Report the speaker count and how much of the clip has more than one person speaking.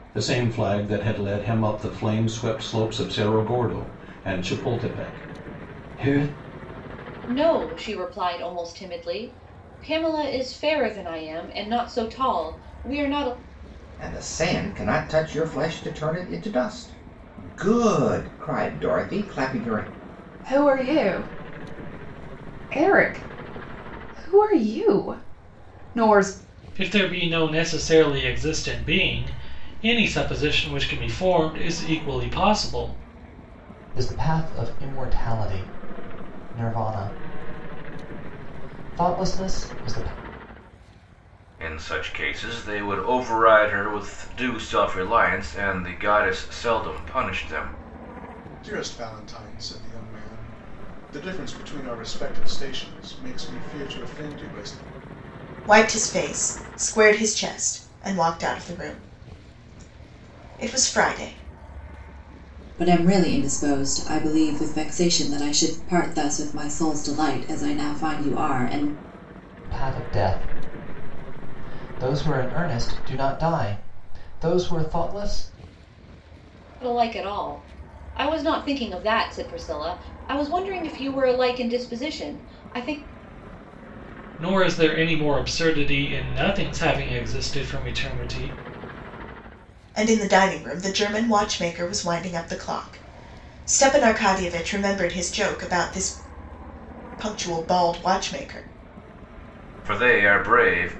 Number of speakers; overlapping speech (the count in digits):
10, no overlap